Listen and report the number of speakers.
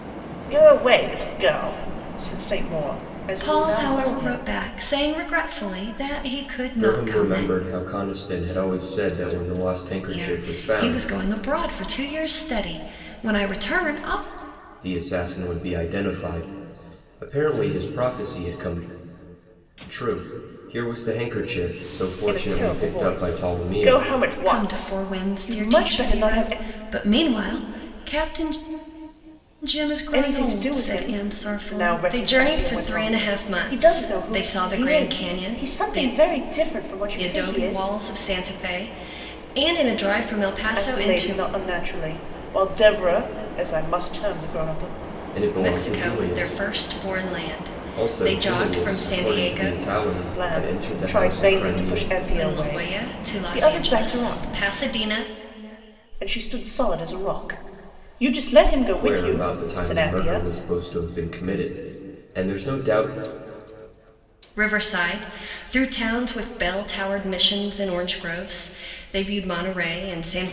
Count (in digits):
3